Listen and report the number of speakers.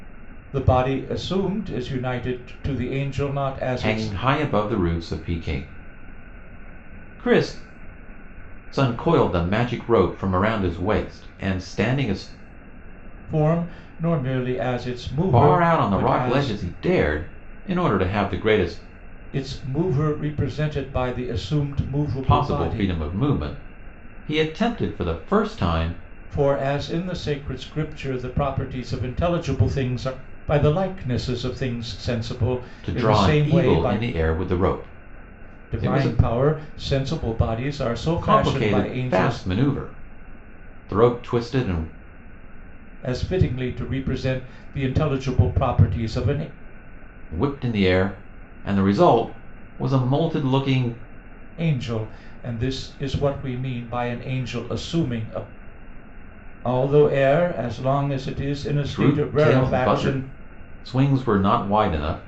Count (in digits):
2